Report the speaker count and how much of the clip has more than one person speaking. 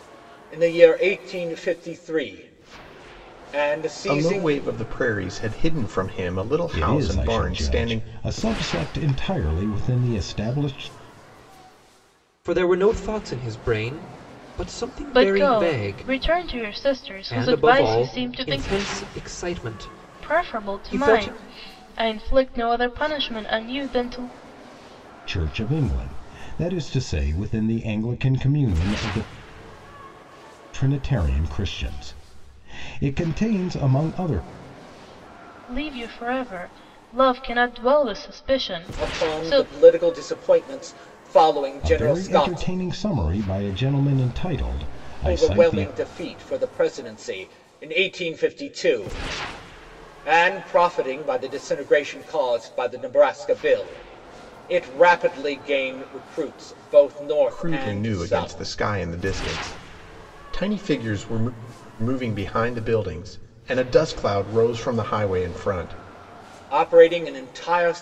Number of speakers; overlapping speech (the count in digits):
5, about 13%